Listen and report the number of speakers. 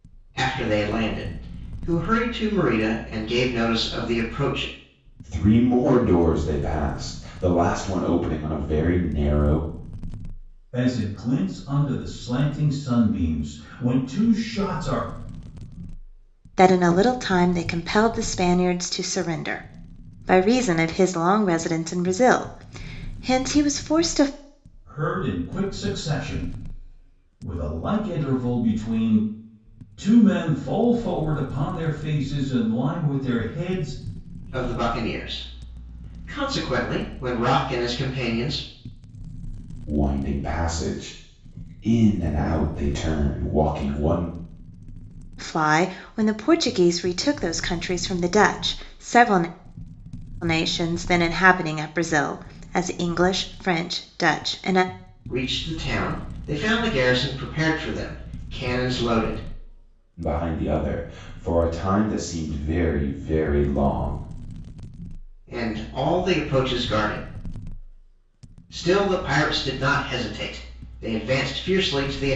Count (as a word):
four